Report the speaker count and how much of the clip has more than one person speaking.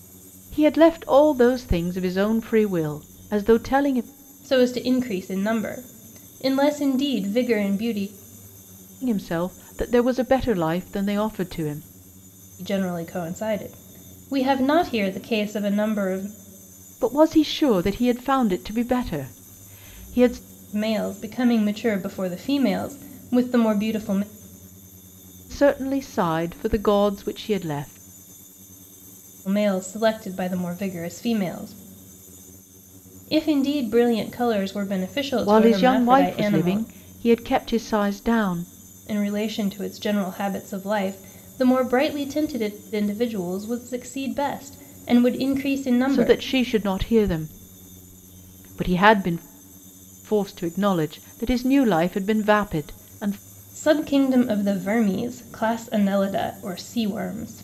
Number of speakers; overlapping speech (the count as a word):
two, about 3%